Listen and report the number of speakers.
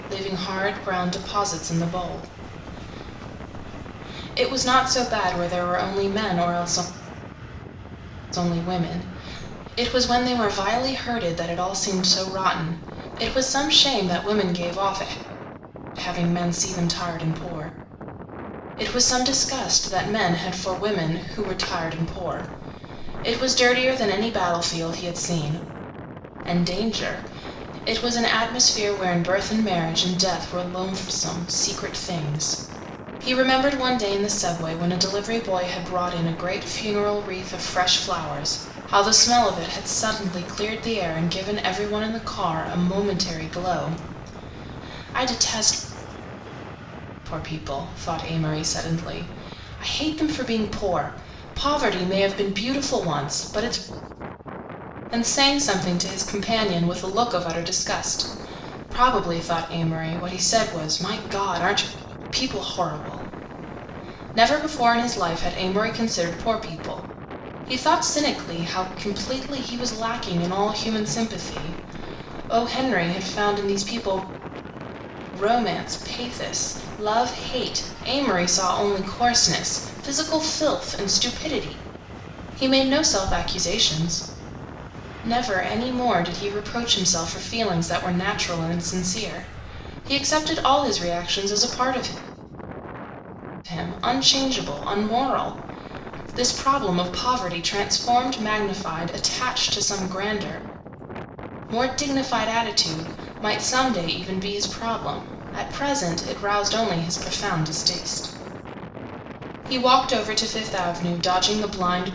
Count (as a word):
one